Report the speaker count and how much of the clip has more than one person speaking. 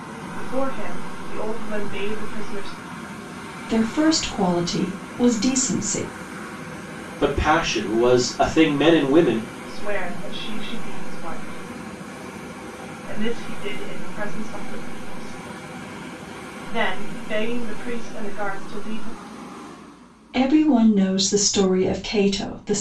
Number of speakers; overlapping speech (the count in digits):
3, no overlap